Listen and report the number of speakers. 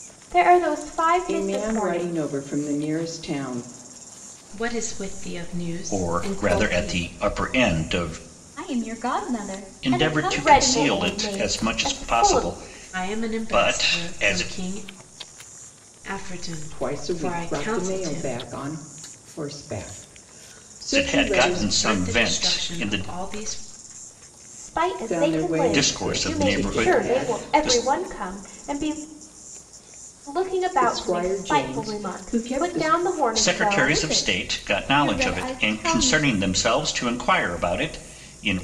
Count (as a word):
five